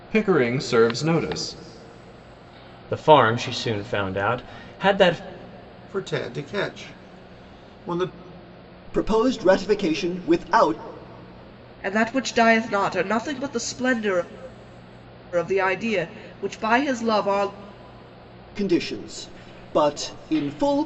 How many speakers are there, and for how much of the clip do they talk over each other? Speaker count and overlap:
5, no overlap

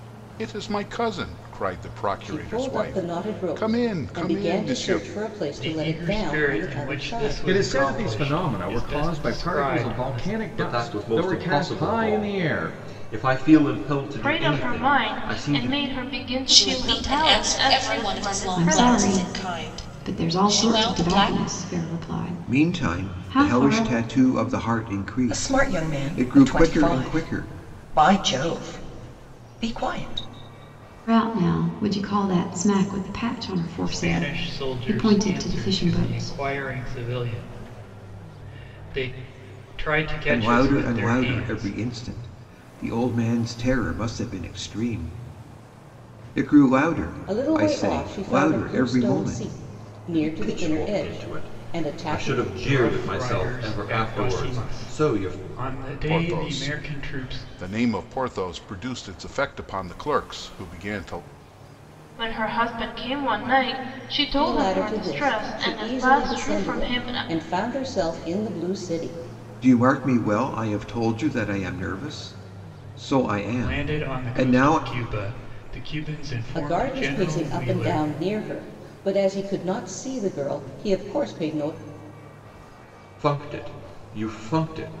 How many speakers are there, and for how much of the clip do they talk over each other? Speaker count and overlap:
10, about 46%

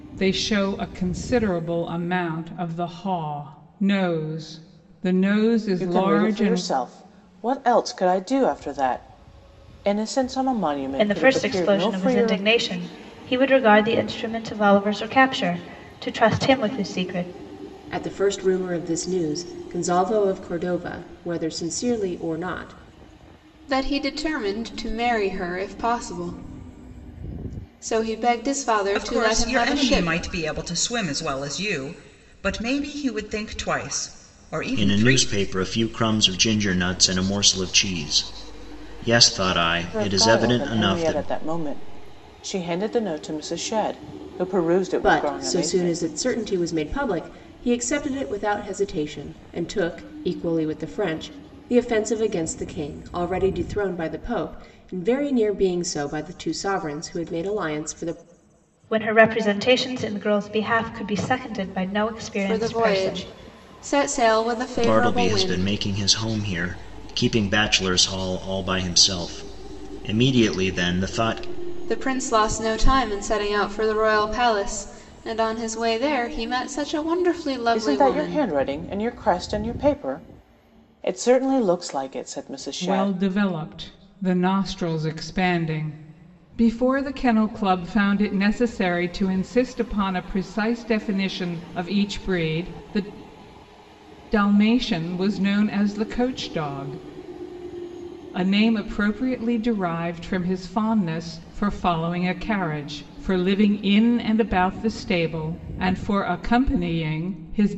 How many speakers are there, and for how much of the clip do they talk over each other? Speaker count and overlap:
7, about 9%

